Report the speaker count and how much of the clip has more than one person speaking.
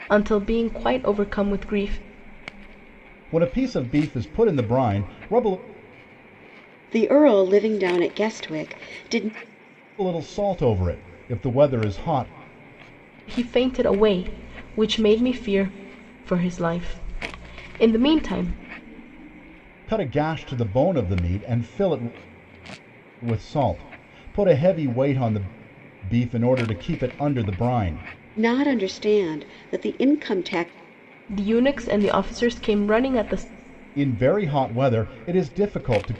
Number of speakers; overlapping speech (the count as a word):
three, no overlap